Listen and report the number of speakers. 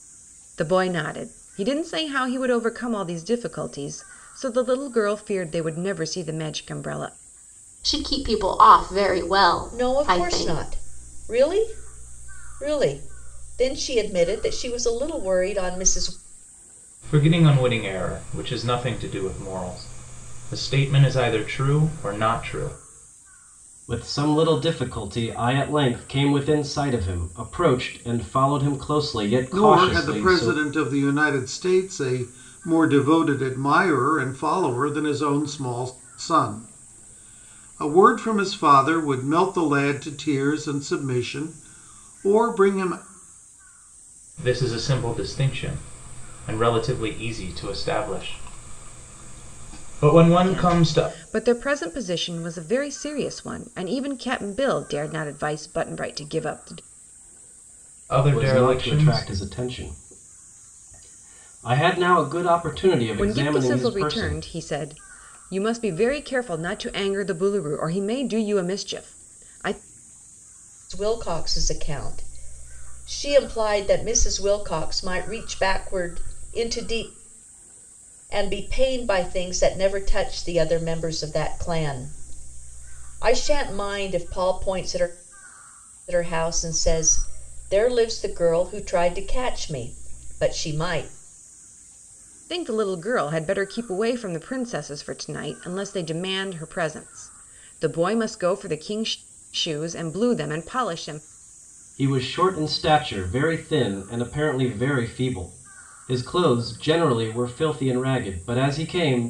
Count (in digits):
6